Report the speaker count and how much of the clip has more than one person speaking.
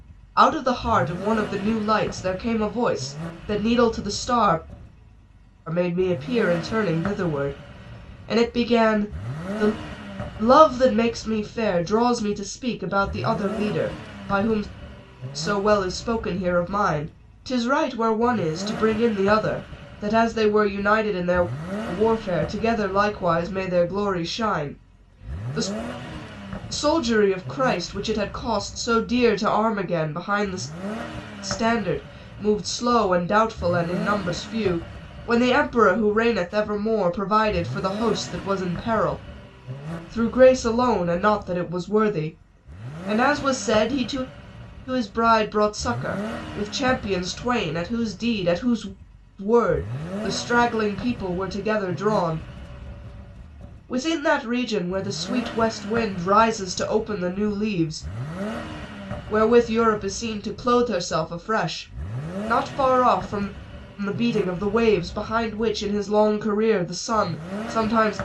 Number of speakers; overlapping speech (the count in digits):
1, no overlap